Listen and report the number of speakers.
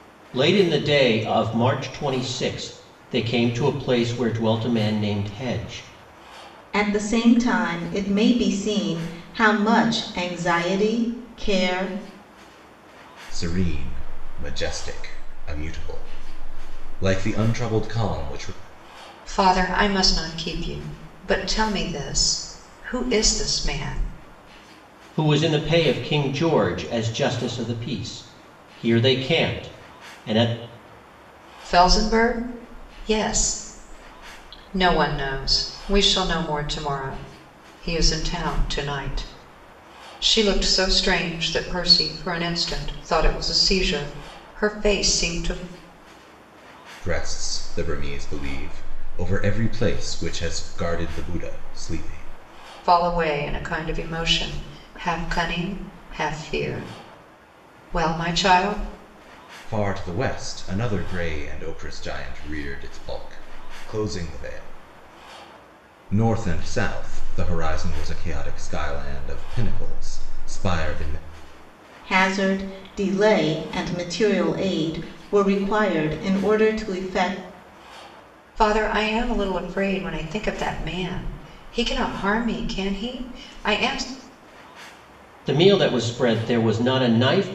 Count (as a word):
four